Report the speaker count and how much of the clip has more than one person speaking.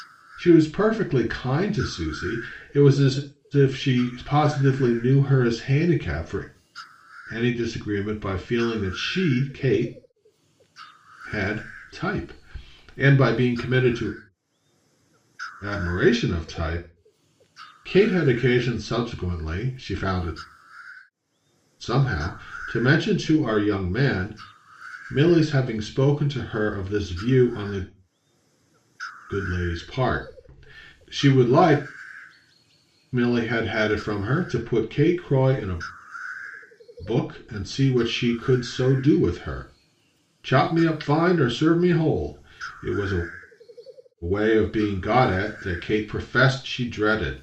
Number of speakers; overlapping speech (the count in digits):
1, no overlap